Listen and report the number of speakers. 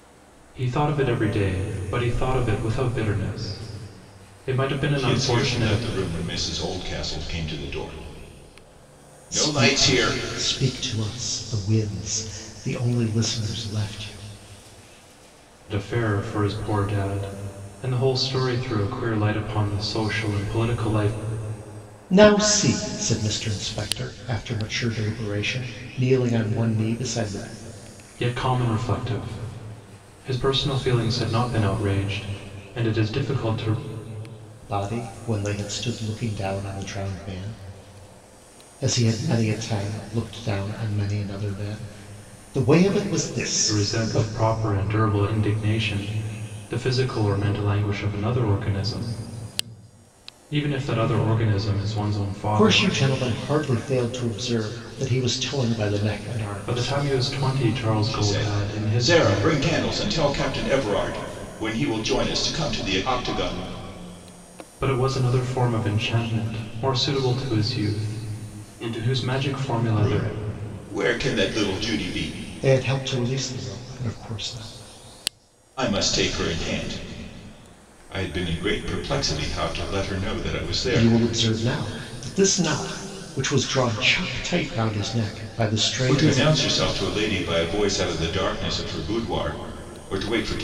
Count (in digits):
3